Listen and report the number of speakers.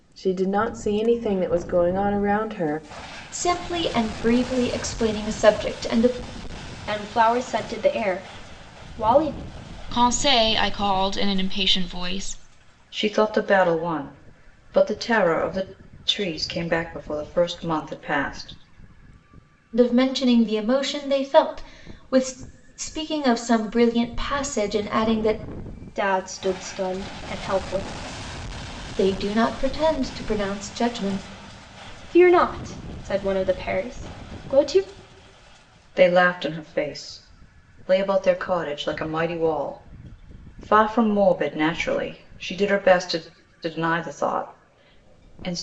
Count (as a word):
five